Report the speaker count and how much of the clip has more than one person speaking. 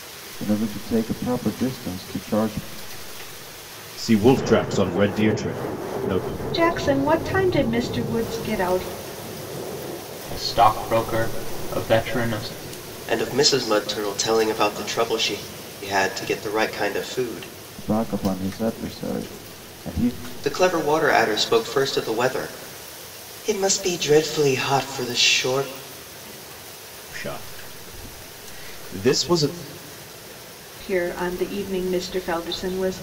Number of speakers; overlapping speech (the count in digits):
5, no overlap